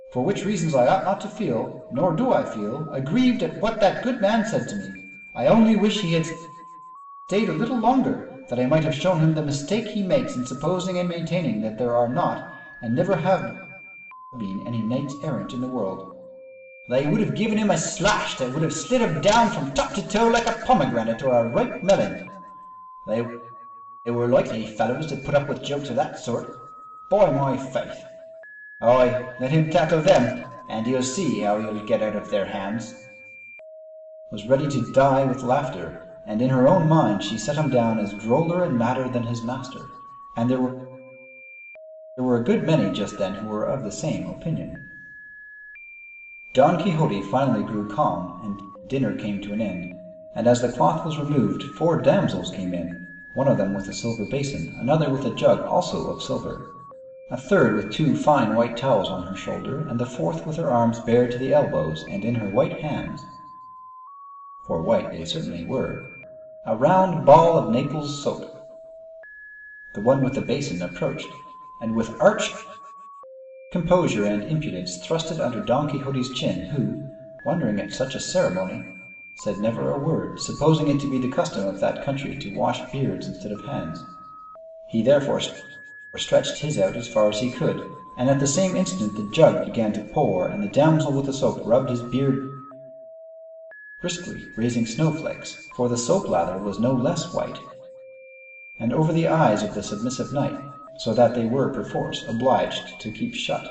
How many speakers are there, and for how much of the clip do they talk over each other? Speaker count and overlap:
1, no overlap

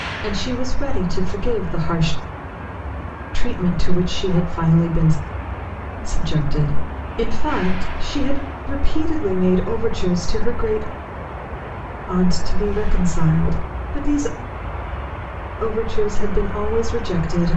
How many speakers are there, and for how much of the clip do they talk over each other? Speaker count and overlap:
1, no overlap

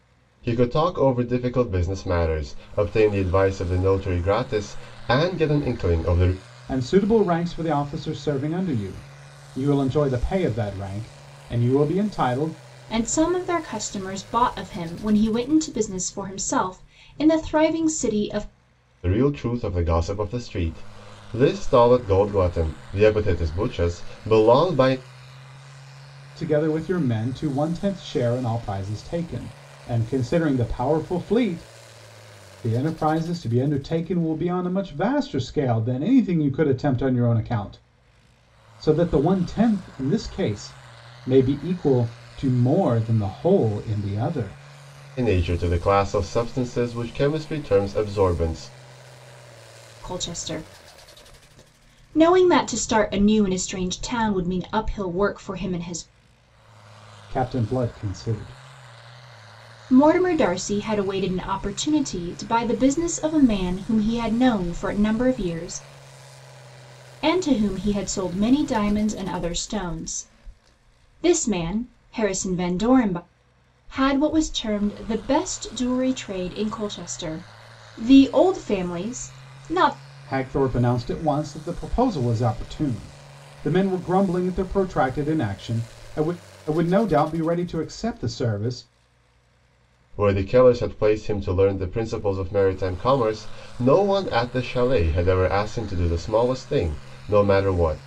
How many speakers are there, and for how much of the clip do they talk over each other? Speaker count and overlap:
3, no overlap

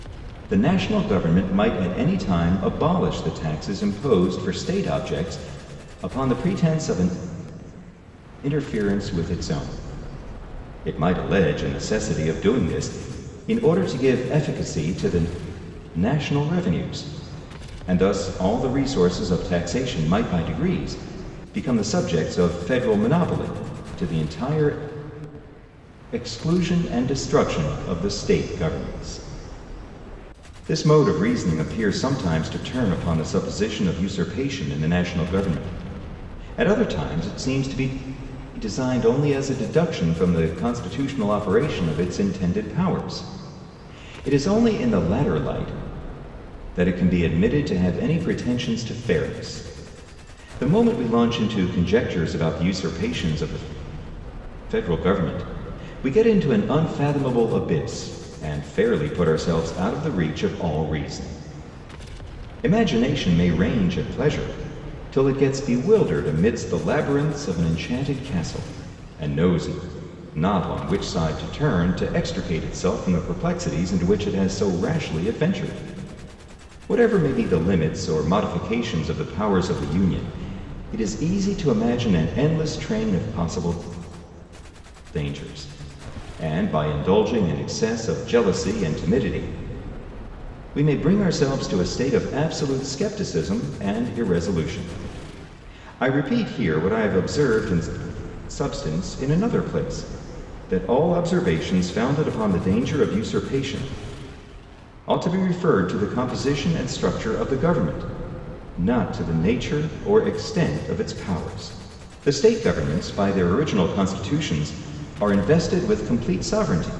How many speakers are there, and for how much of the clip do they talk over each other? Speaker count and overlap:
1, no overlap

